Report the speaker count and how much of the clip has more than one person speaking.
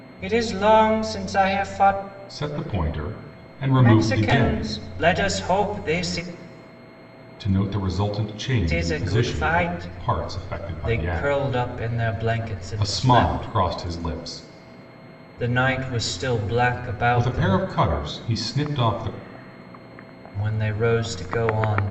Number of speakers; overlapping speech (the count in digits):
2, about 22%